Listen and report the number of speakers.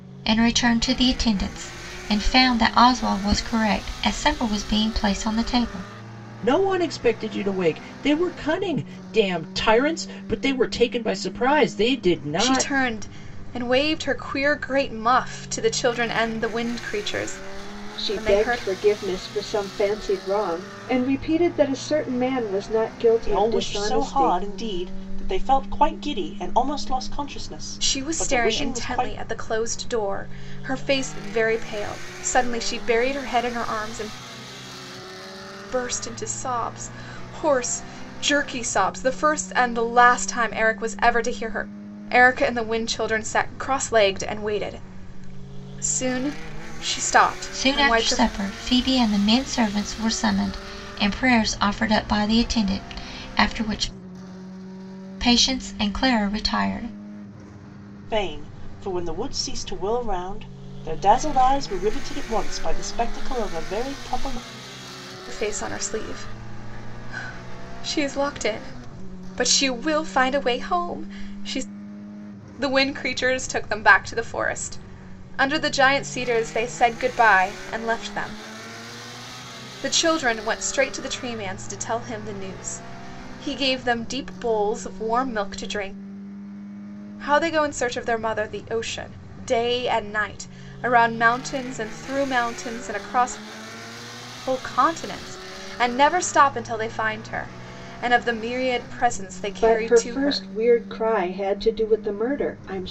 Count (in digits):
5